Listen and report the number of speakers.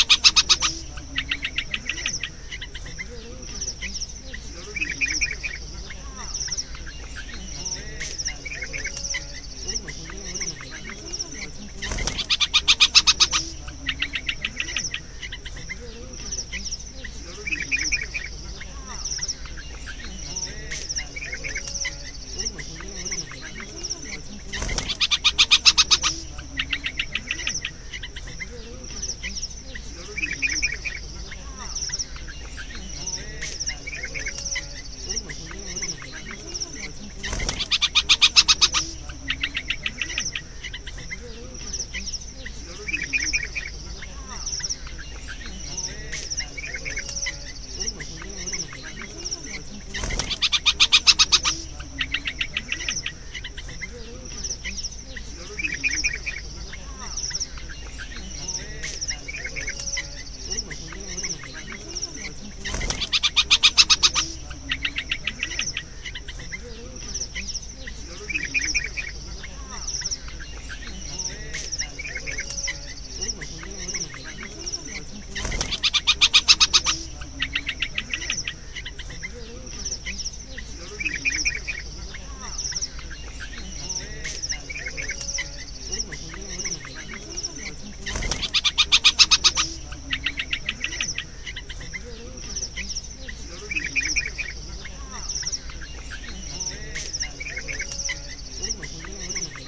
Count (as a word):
zero